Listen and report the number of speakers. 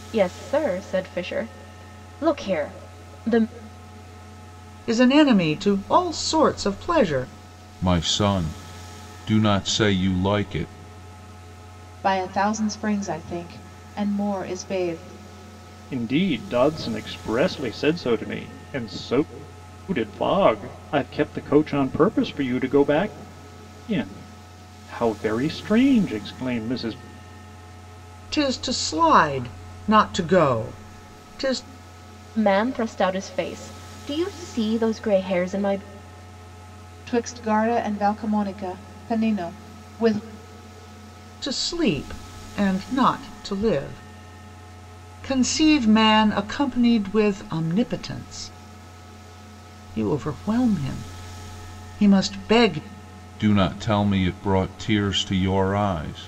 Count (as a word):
five